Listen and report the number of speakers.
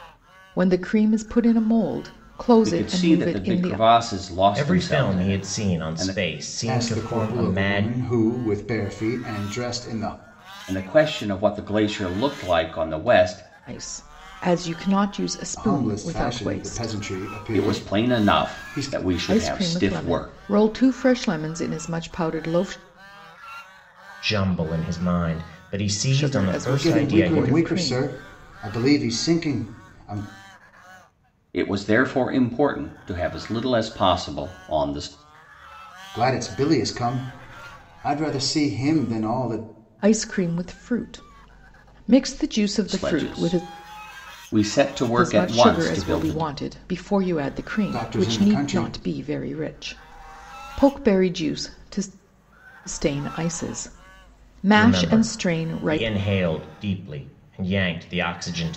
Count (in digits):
4